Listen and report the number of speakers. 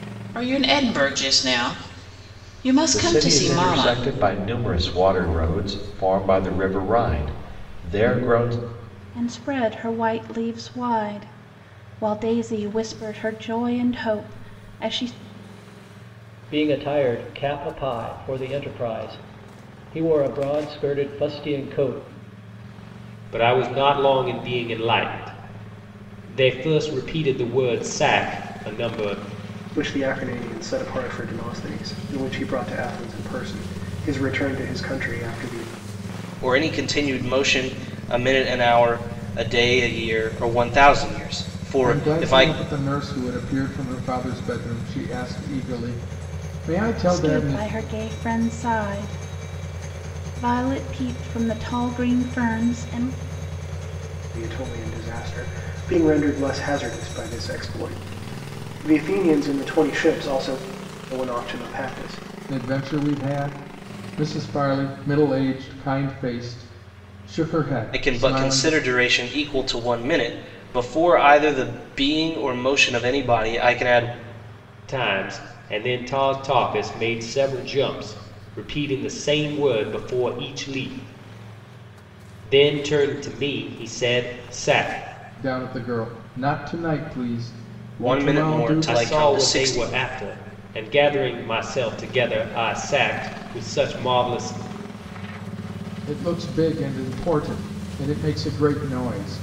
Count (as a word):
eight